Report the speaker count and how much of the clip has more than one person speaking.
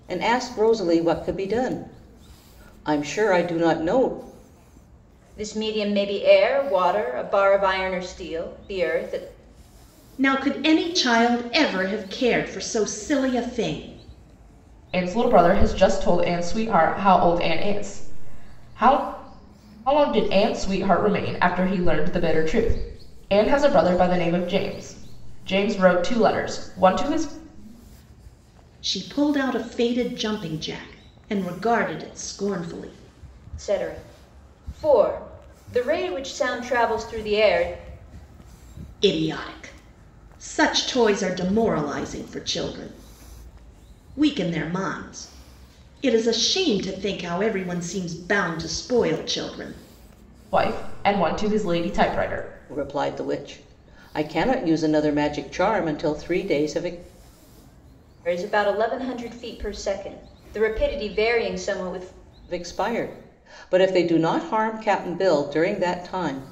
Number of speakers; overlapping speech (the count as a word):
four, no overlap